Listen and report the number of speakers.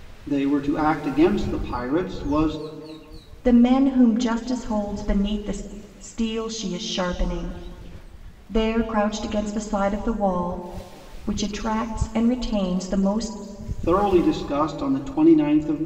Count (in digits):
2